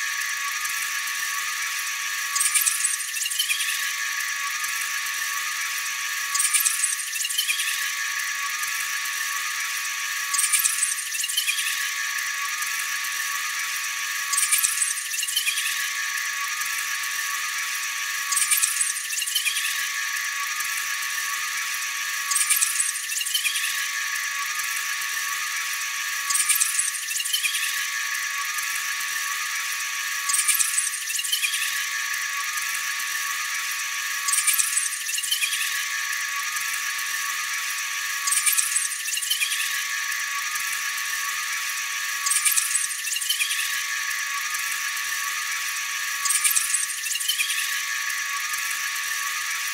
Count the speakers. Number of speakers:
0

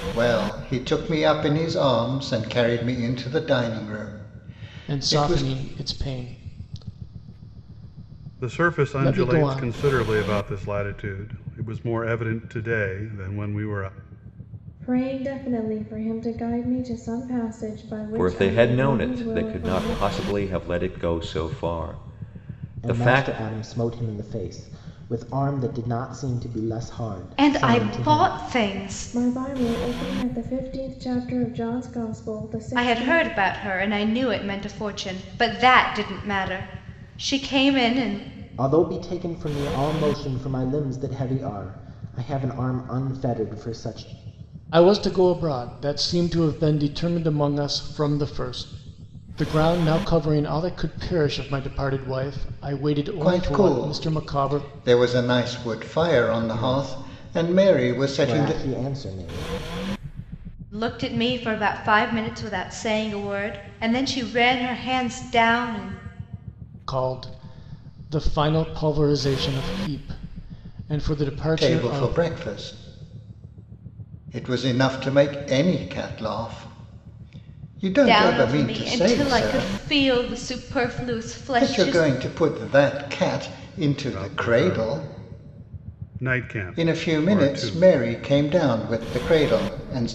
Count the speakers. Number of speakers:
7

